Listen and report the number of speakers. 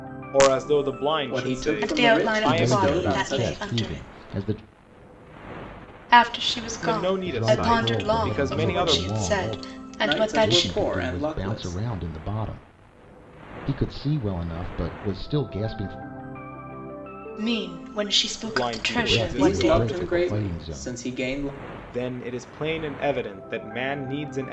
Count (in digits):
4